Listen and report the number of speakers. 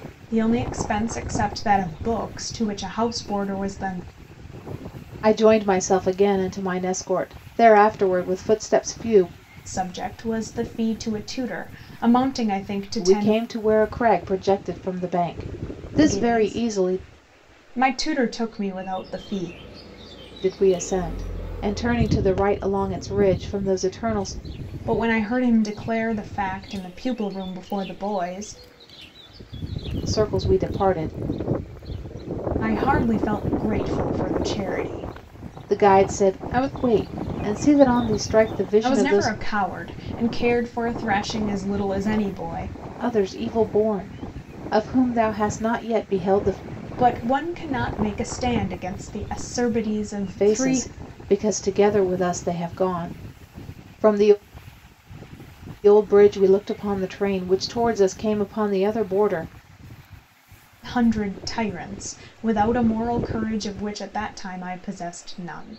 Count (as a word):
two